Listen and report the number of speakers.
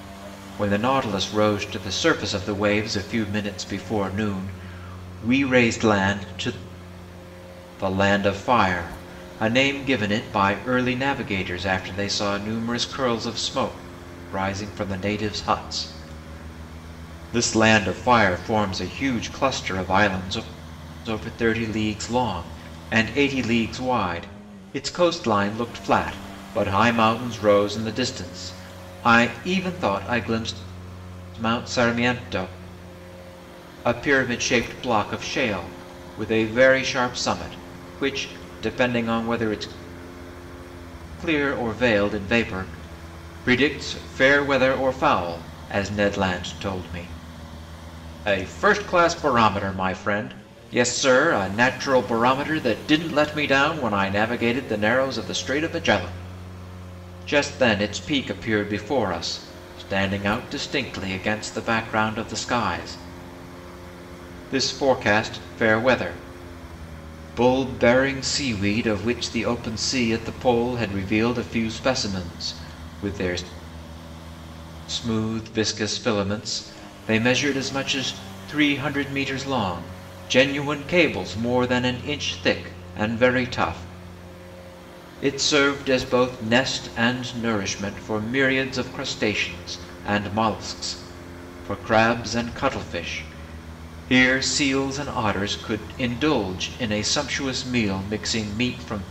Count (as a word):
one